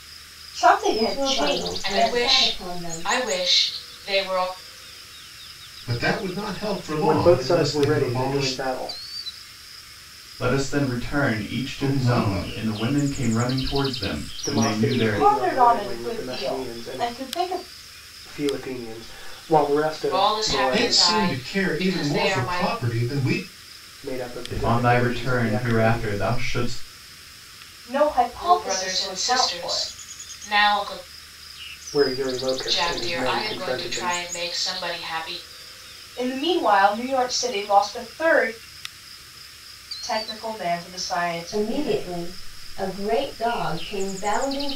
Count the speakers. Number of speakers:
6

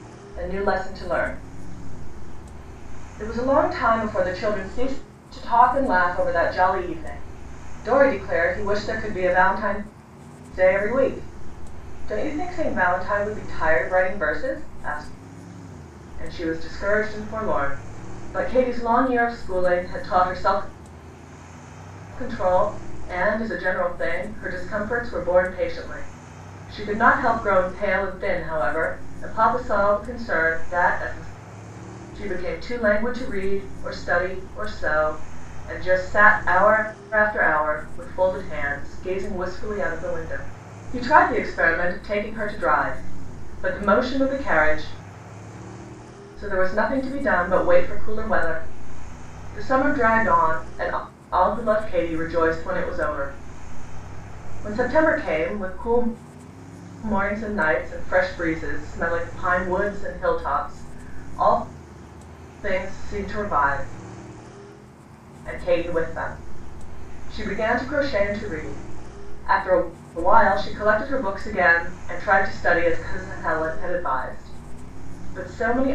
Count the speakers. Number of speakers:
1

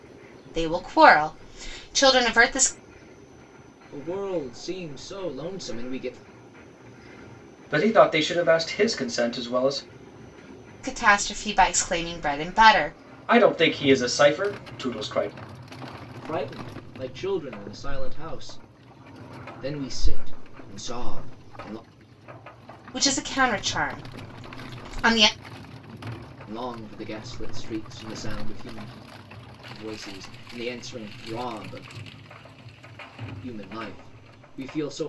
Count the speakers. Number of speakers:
3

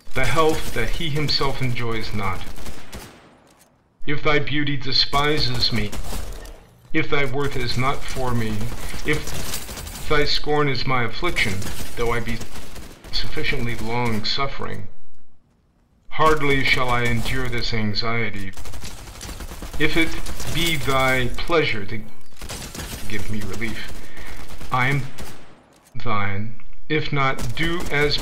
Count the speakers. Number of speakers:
1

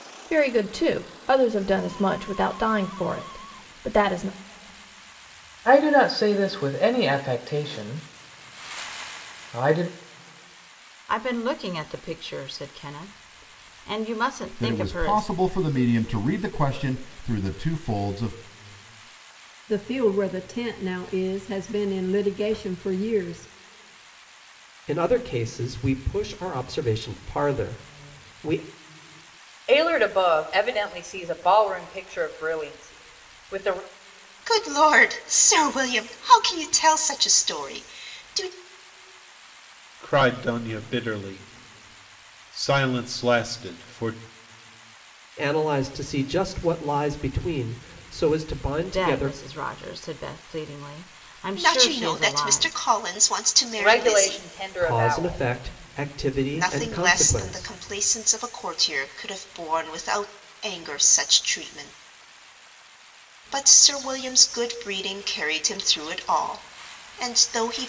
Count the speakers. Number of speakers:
9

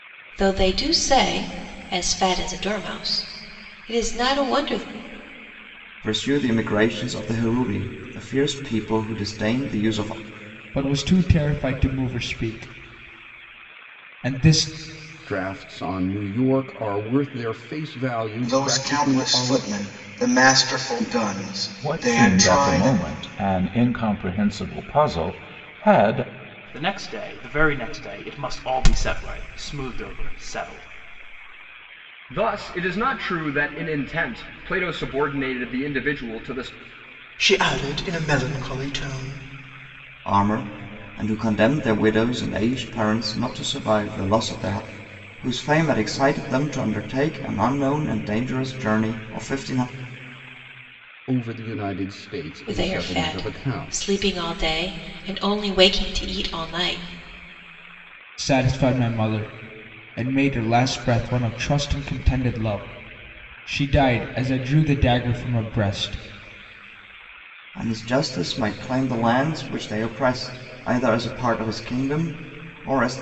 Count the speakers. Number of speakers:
9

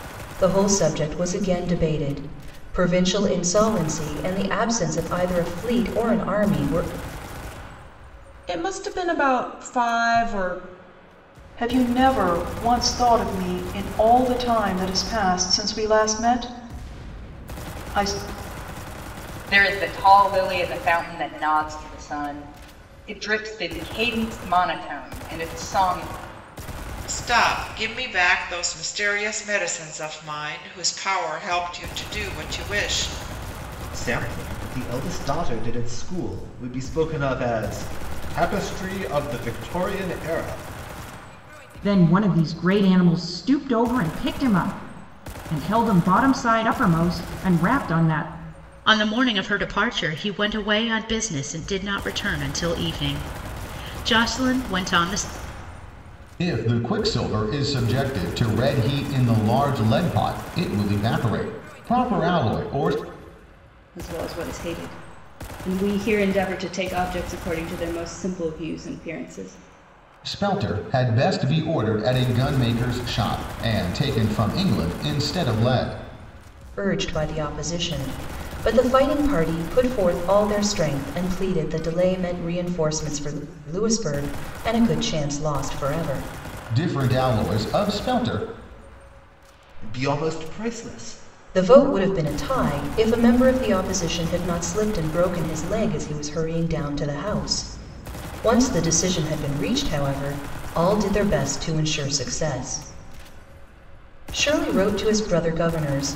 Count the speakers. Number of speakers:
10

